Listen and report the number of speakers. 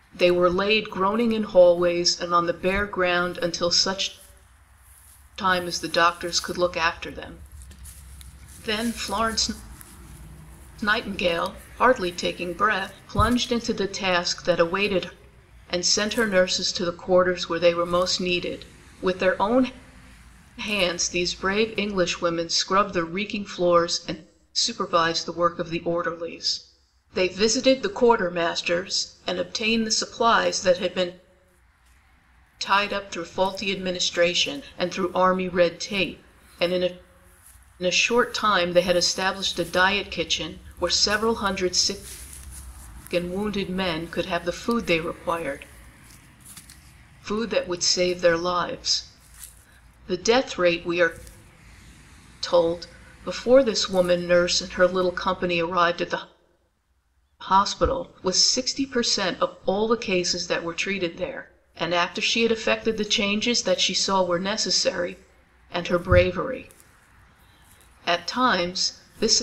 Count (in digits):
1